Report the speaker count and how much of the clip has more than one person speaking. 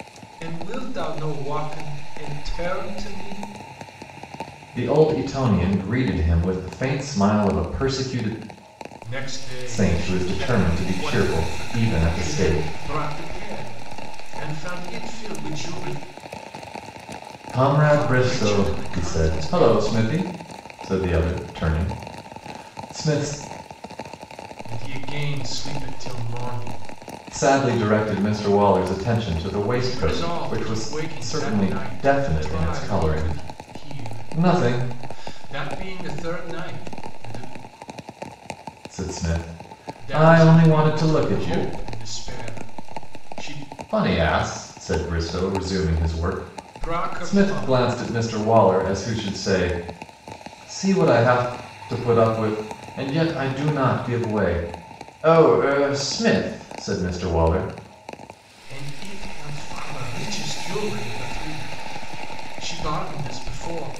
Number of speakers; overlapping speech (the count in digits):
2, about 20%